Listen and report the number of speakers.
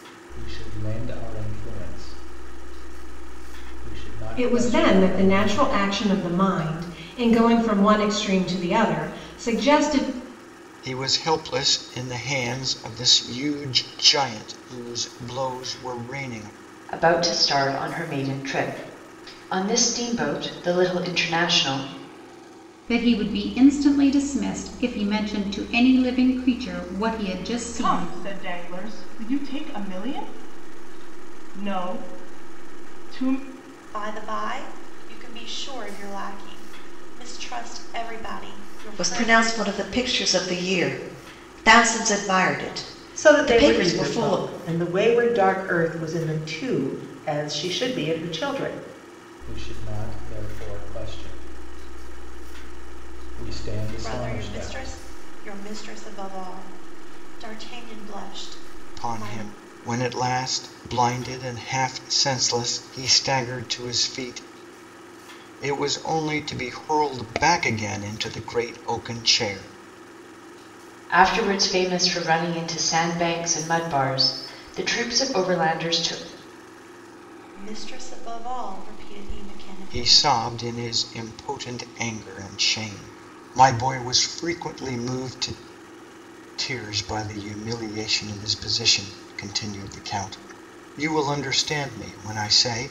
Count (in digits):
9